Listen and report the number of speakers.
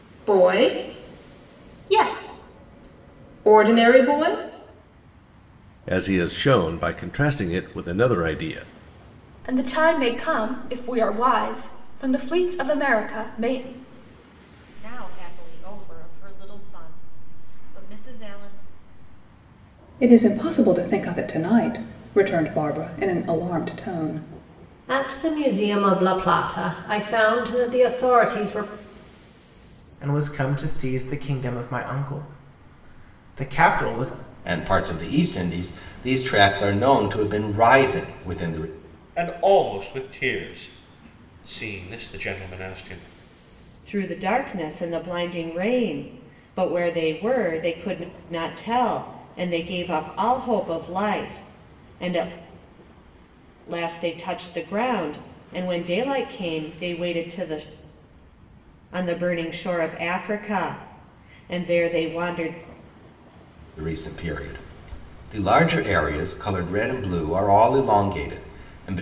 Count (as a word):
ten